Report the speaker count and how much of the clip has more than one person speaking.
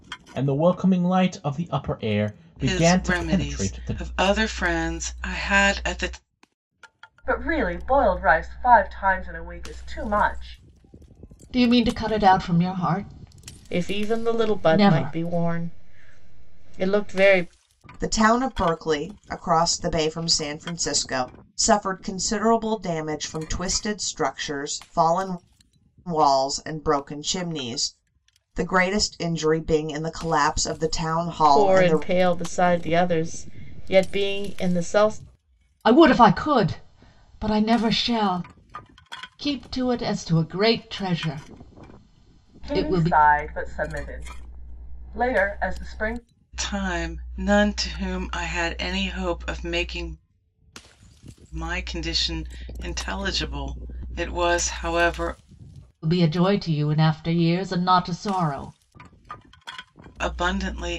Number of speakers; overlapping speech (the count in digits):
6, about 7%